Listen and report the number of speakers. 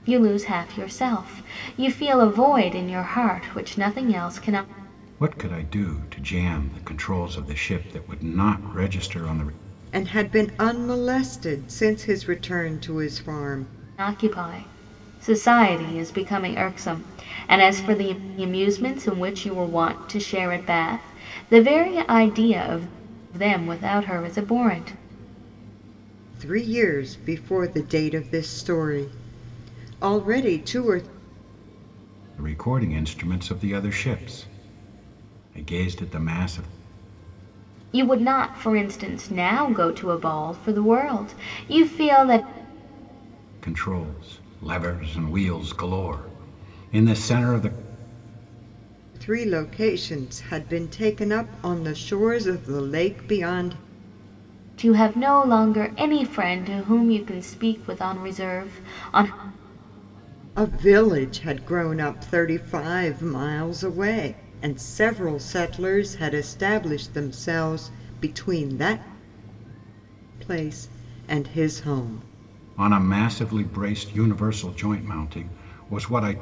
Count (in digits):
3